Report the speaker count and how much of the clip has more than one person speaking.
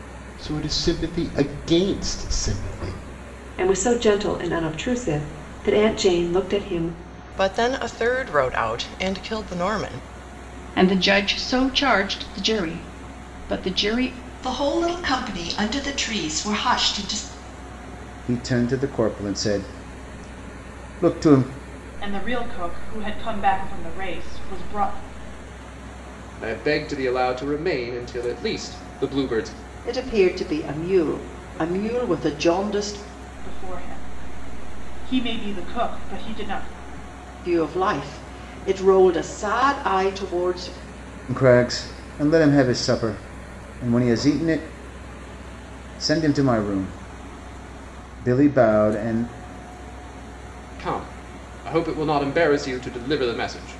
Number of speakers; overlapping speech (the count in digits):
9, no overlap